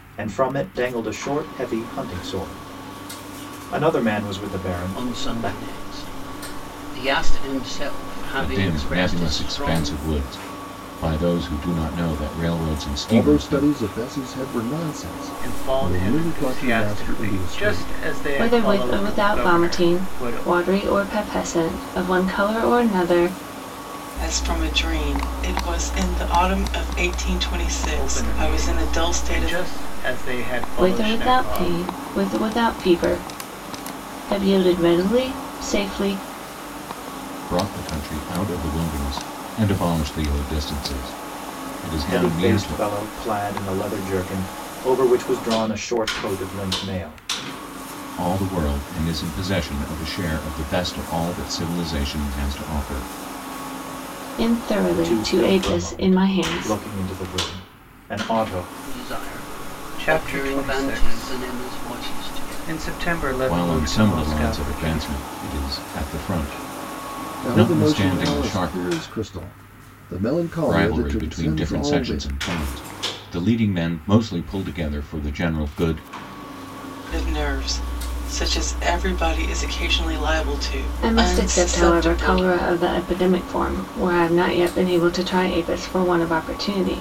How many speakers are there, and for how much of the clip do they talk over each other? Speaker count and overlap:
7, about 26%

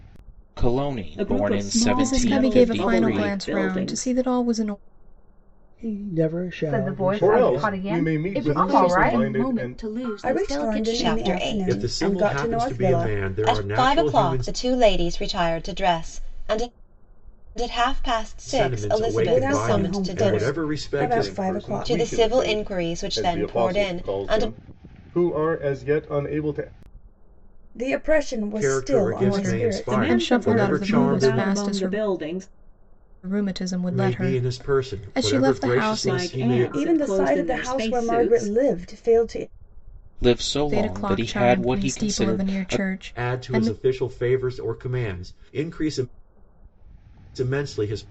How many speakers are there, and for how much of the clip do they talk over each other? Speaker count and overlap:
10, about 57%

